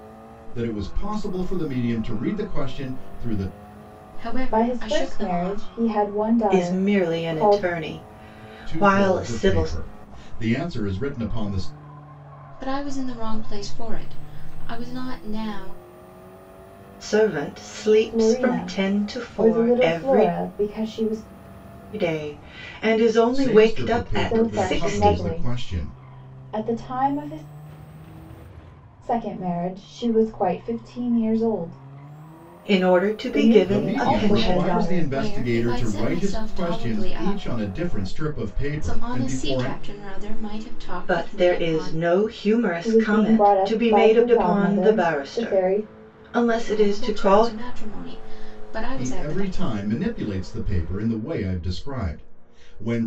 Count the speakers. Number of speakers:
4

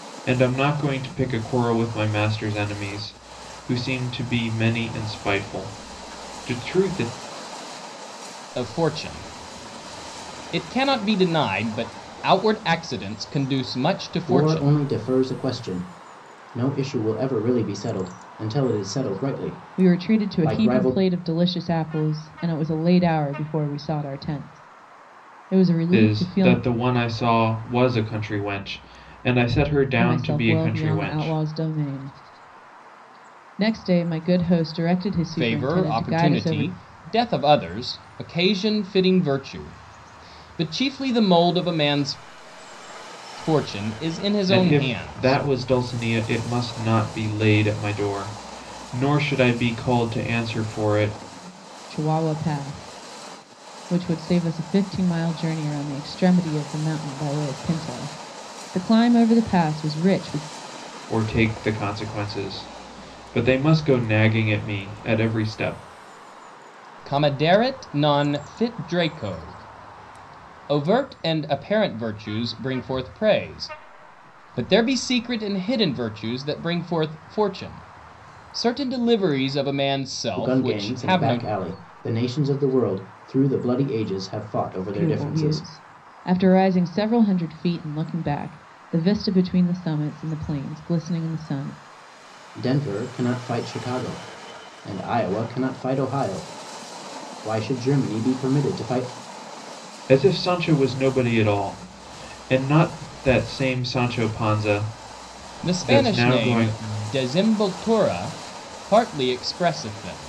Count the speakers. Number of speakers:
4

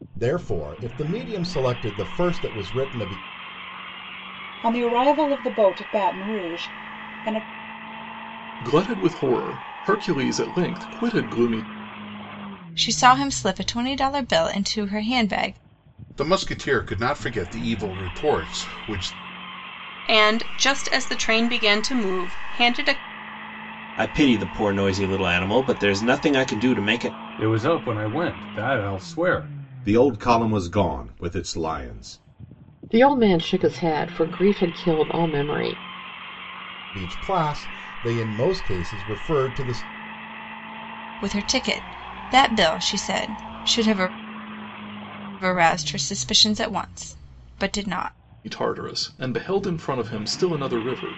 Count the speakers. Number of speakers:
10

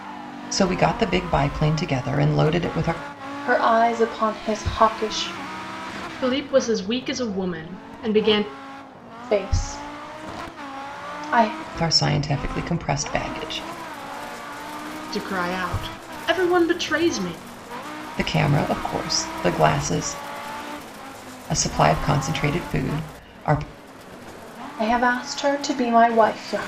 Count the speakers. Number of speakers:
3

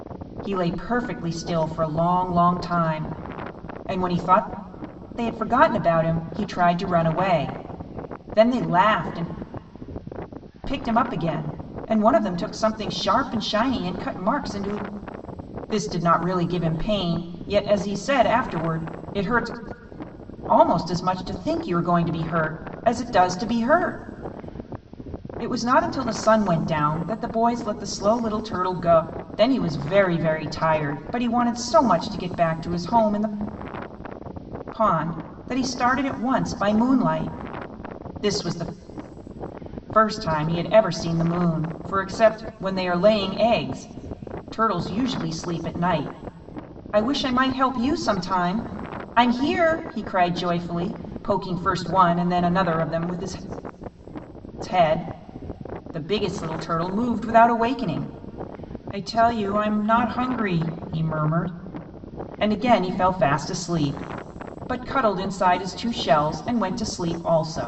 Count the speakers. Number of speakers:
1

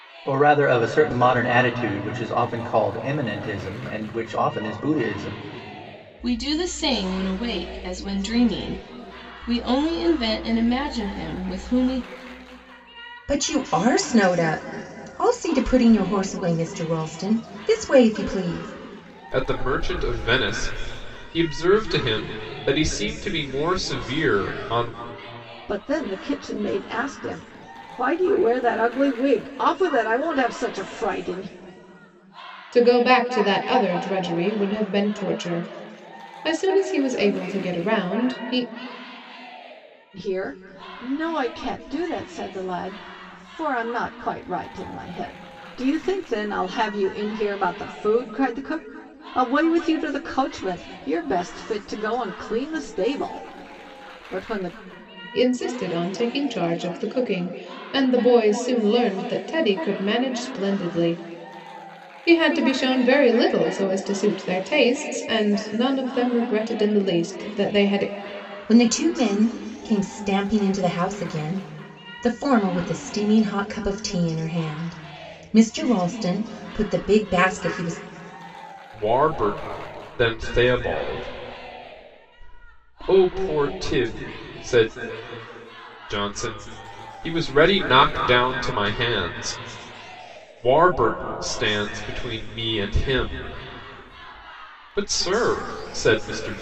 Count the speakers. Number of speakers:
6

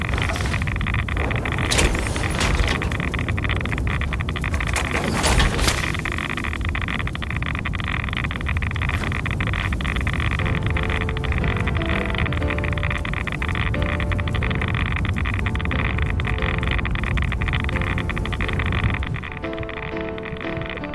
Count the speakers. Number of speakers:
0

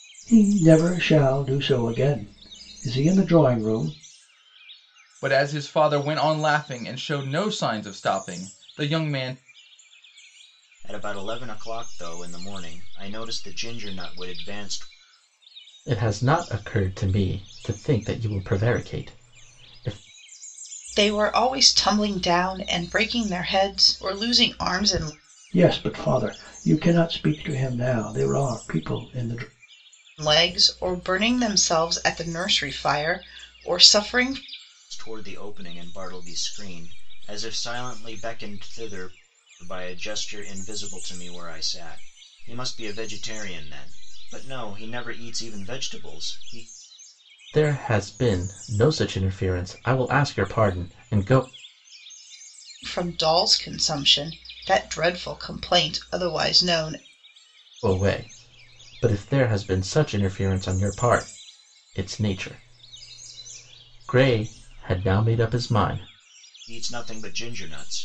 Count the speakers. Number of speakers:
5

